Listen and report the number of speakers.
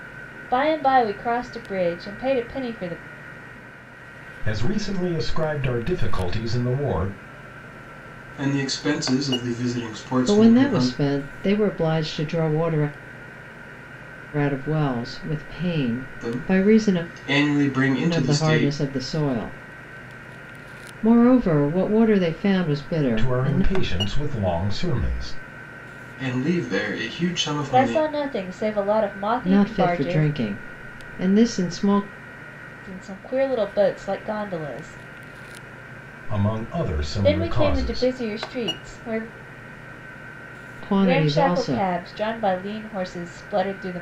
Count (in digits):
4